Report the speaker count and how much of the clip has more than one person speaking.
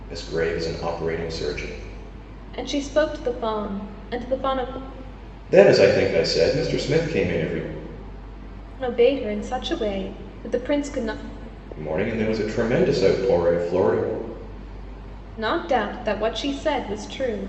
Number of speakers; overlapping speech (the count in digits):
2, no overlap